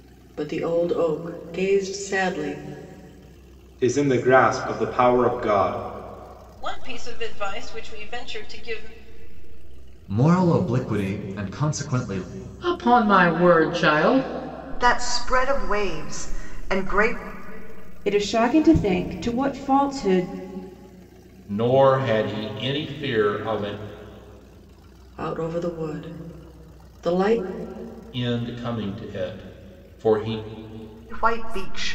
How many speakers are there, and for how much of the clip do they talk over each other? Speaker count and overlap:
8, no overlap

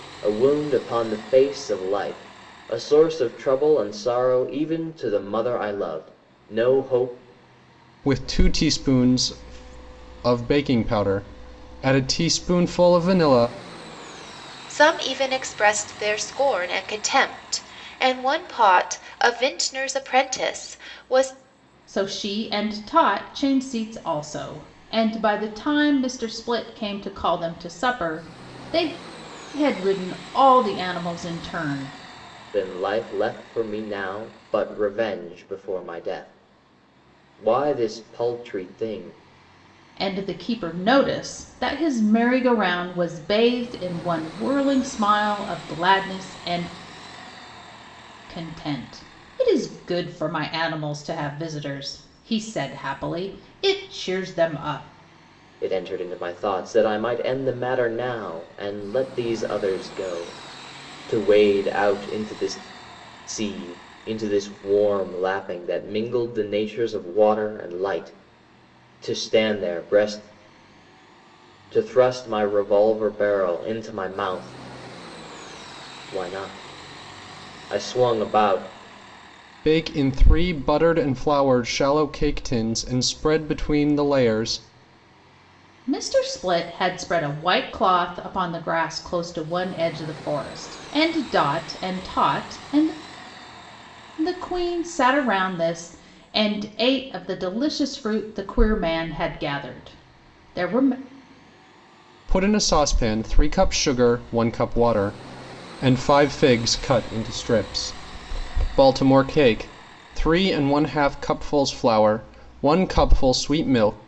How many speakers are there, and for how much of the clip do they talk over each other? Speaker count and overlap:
4, no overlap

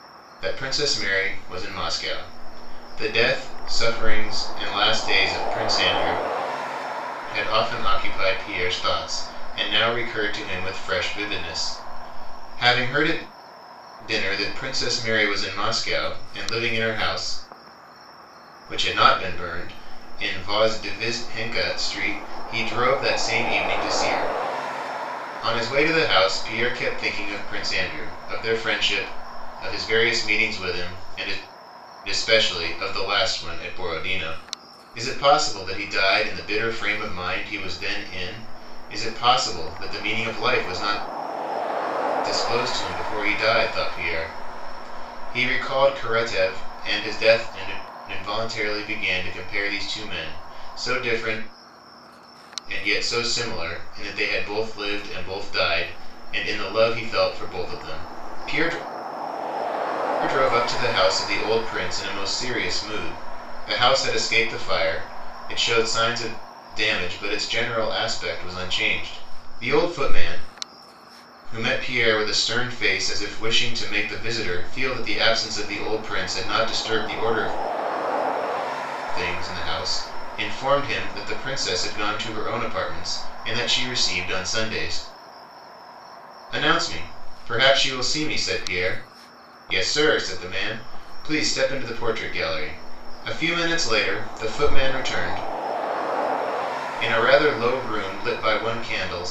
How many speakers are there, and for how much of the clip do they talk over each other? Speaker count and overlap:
1, no overlap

